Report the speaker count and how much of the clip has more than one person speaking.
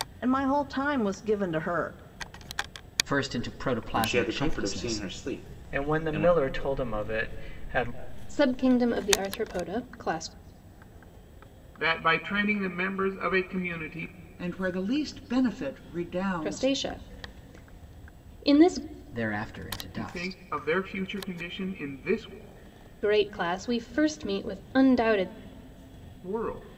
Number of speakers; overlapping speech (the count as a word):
seven, about 10%